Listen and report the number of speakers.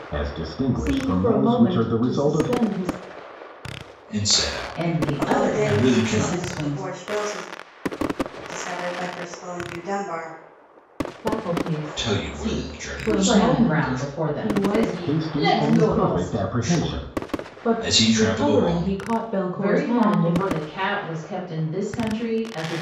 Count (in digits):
5